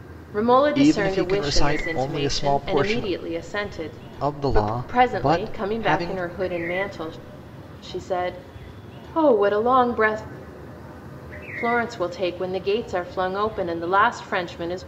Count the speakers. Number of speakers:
2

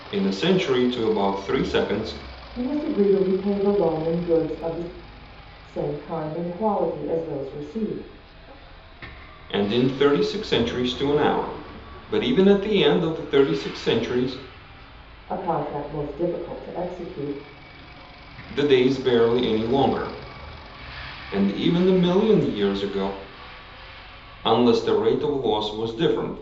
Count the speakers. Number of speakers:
2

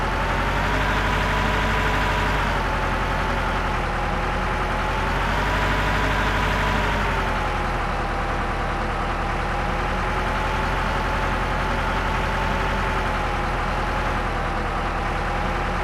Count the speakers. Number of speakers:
0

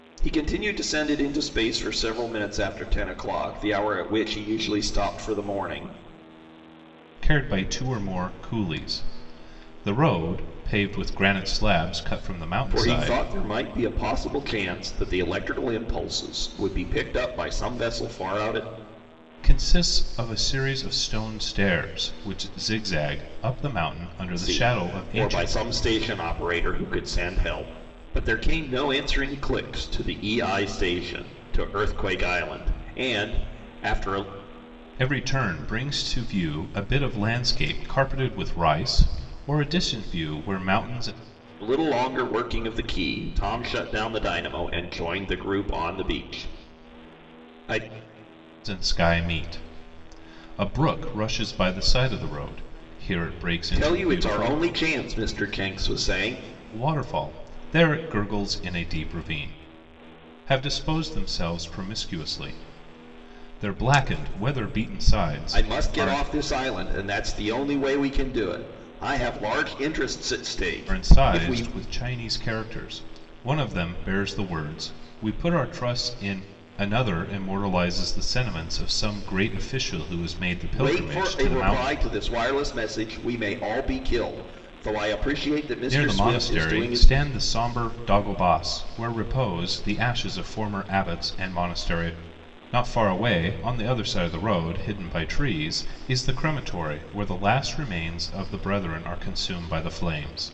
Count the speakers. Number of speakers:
2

